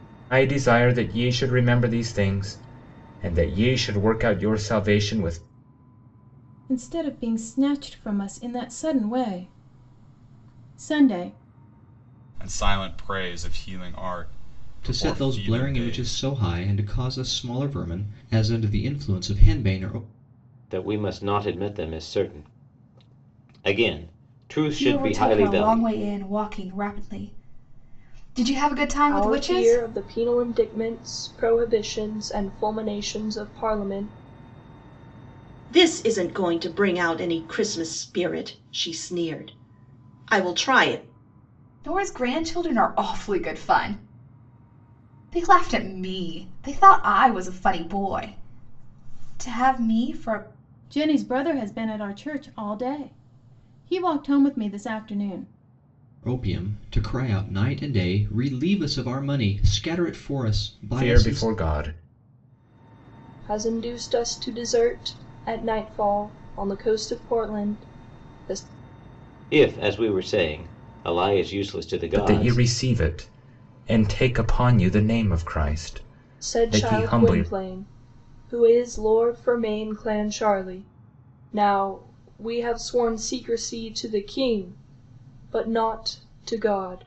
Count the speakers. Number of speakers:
8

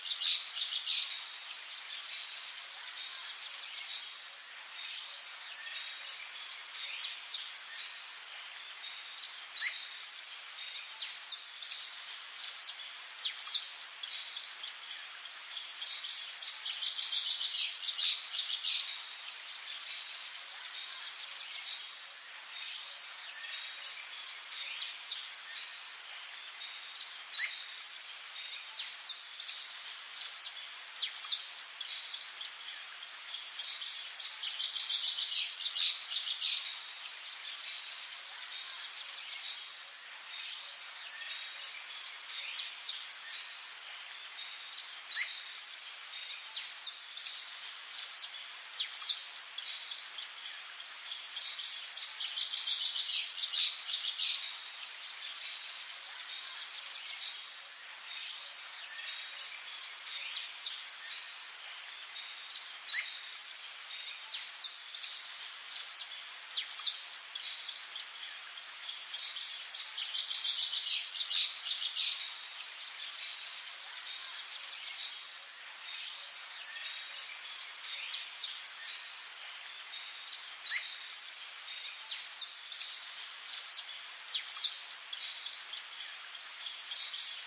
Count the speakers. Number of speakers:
0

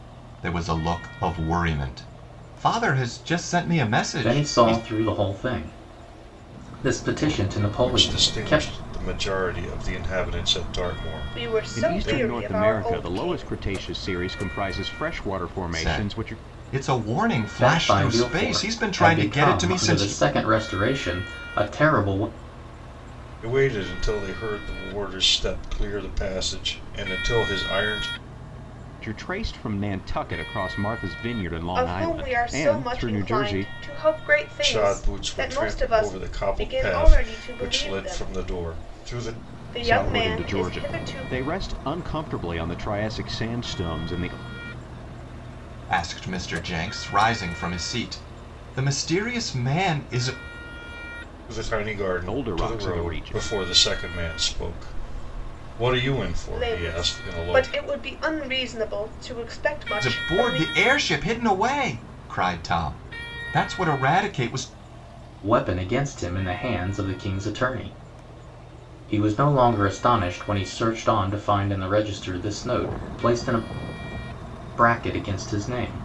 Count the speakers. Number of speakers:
5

